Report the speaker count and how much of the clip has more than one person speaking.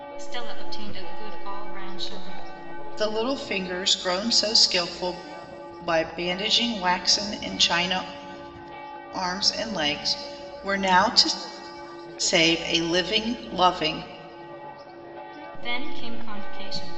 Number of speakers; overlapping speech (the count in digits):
2, no overlap